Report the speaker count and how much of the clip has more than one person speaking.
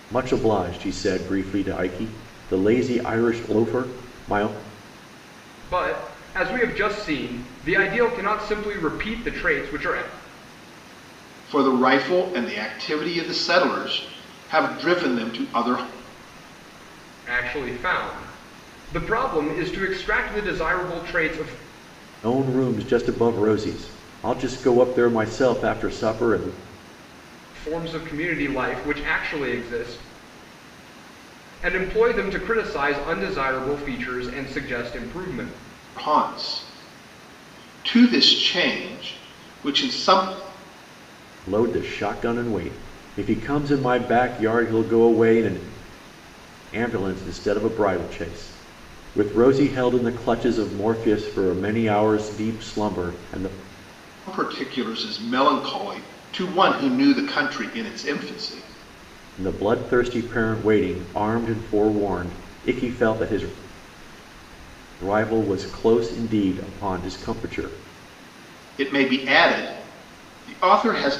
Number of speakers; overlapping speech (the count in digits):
3, no overlap